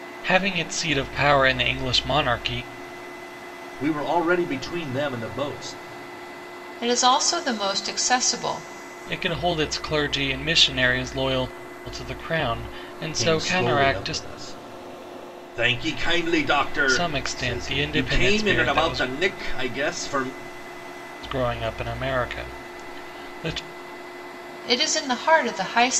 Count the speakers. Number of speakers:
3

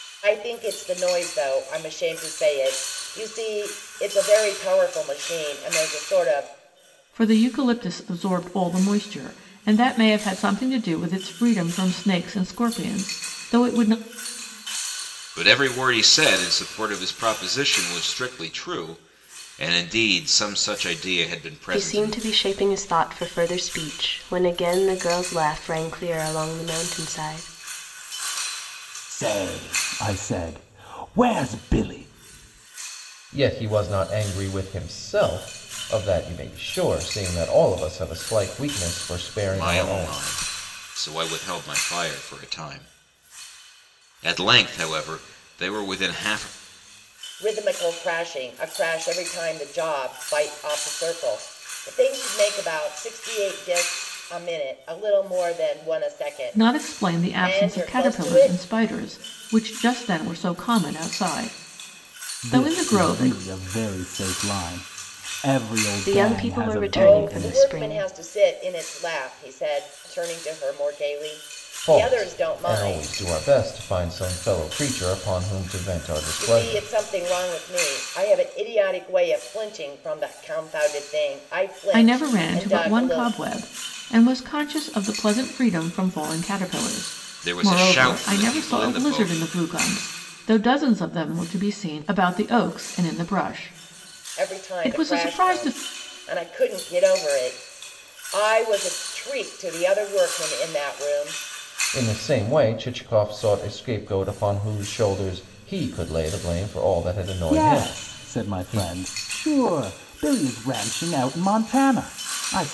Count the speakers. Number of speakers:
6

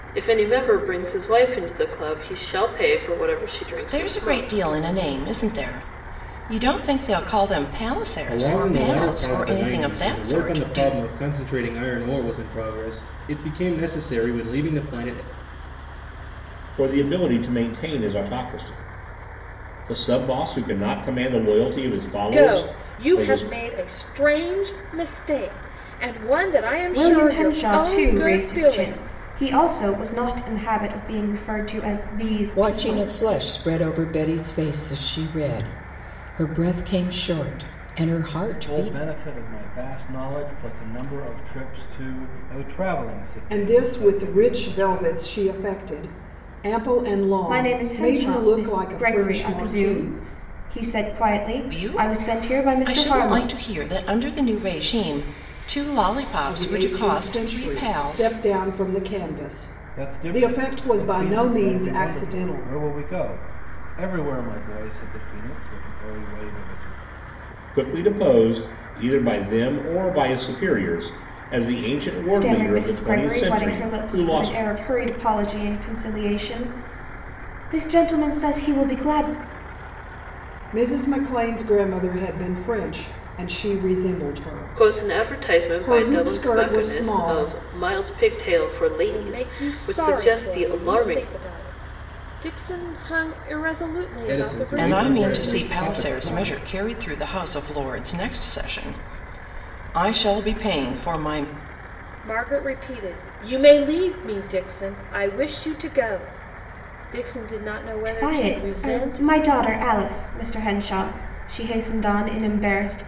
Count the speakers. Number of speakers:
9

